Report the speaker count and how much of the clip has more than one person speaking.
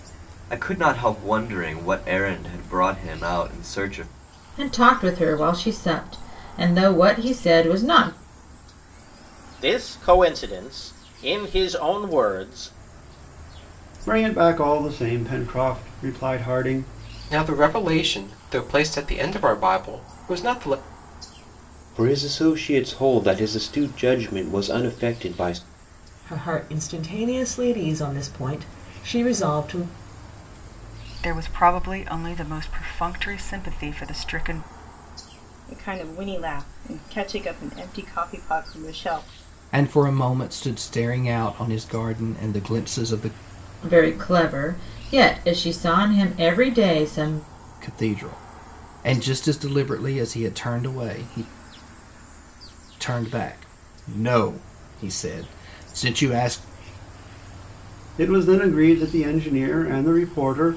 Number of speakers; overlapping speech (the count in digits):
10, no overlap